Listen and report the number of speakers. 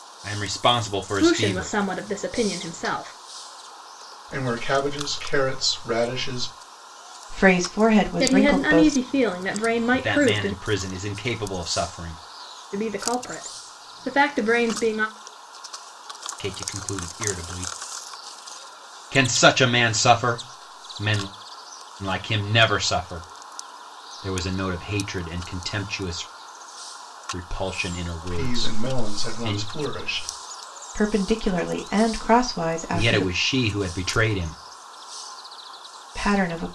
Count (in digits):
4